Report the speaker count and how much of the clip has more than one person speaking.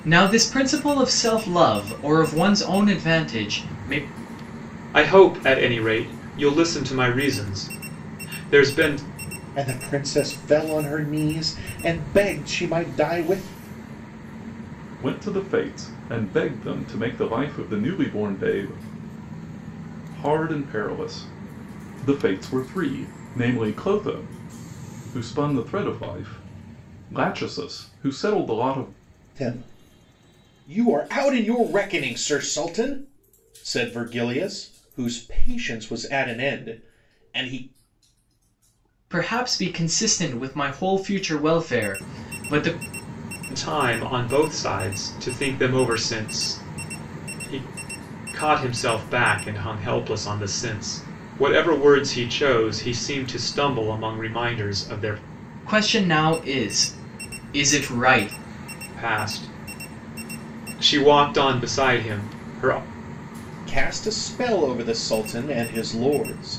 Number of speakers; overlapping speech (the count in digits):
4, no overlap